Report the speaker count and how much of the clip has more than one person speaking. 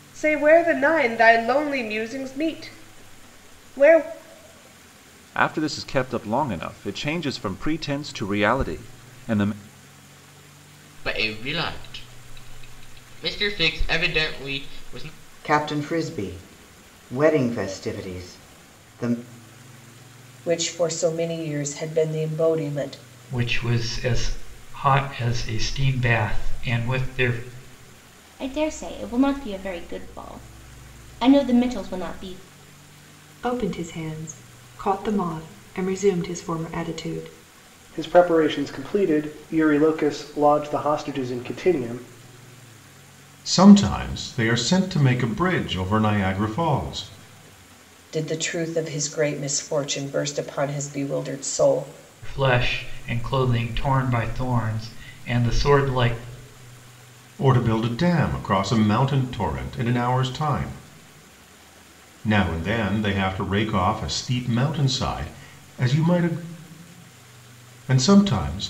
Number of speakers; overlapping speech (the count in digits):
10, no overlap